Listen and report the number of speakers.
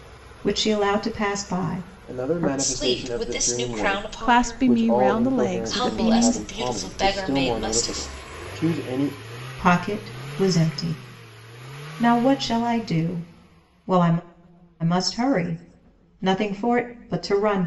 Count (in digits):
4